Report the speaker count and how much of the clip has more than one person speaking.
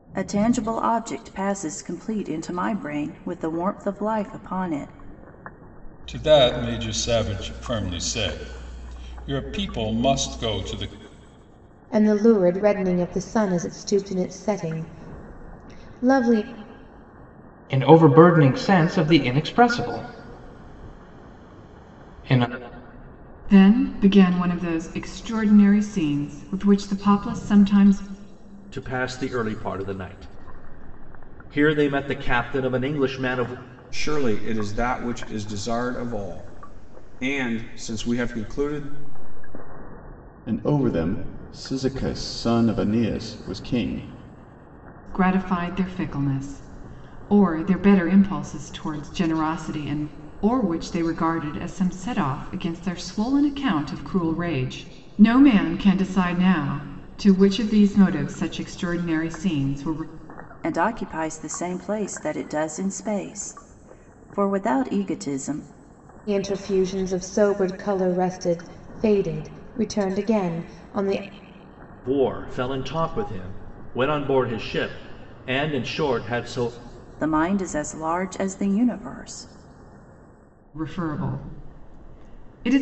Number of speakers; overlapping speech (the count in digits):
8, no overlap